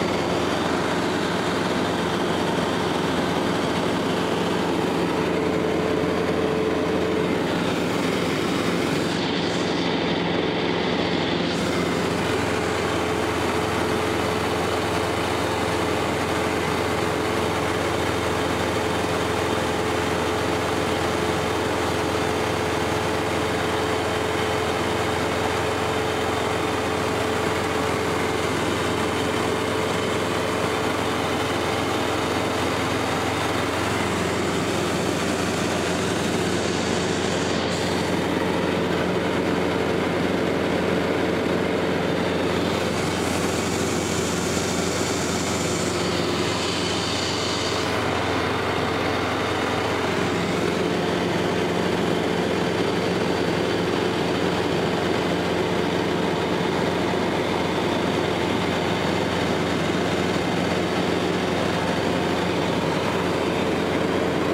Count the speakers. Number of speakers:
zero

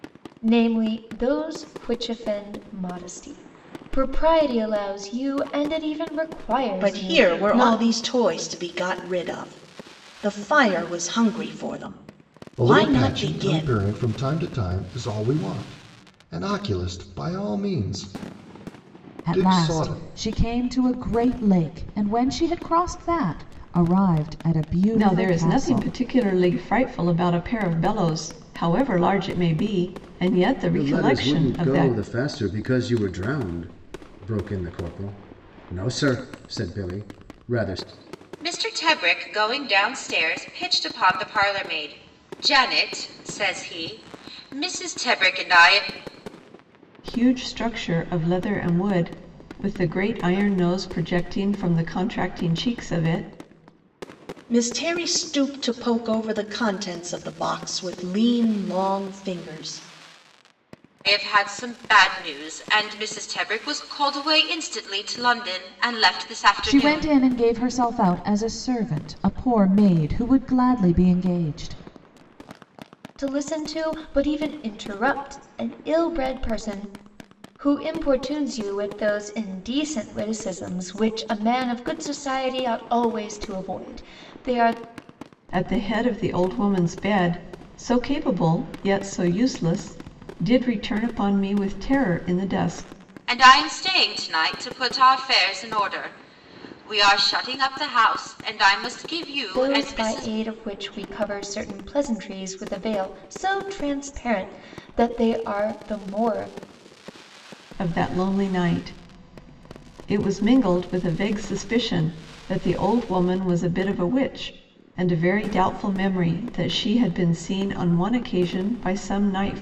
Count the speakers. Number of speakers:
seven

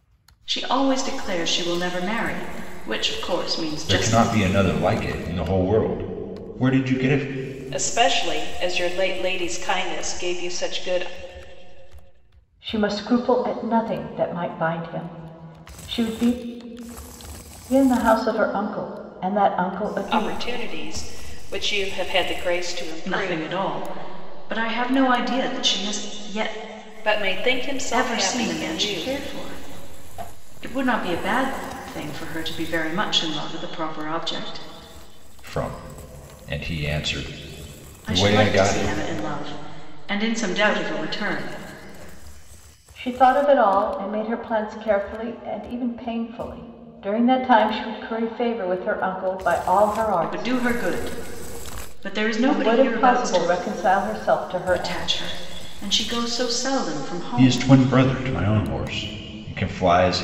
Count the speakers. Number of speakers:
four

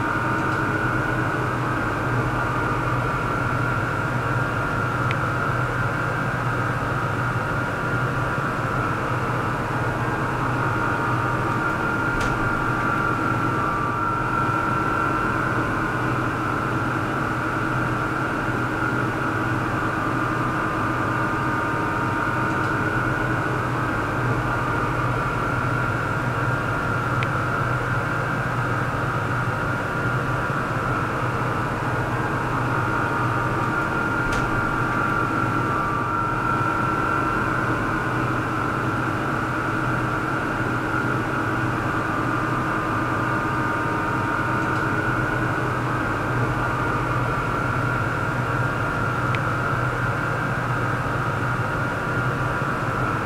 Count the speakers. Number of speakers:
zero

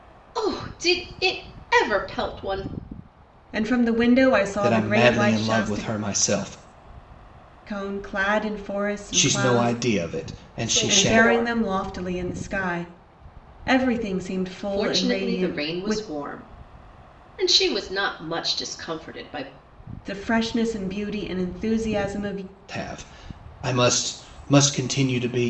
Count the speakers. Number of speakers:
three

